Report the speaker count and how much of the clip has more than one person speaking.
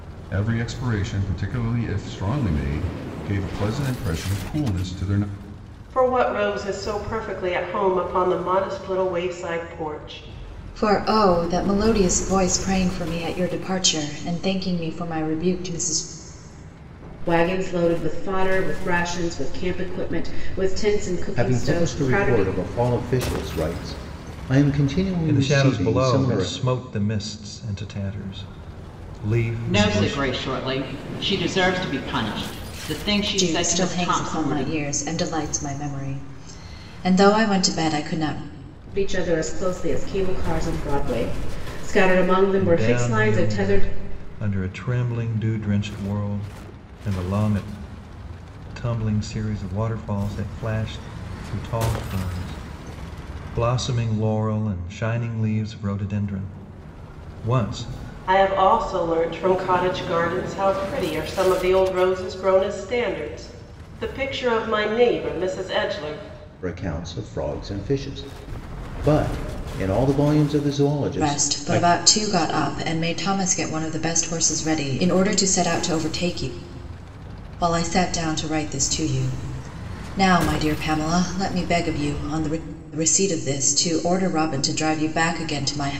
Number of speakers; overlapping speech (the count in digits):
7, about 8%